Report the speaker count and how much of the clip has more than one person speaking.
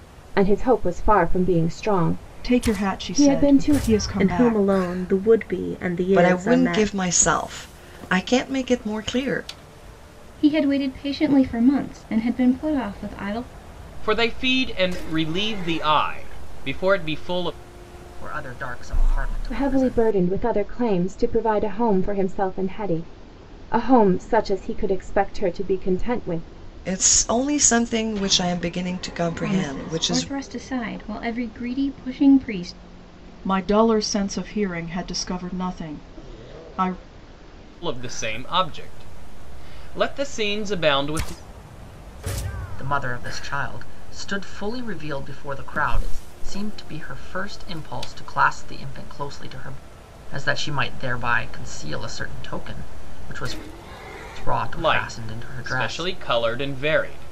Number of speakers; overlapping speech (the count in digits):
7, about 10%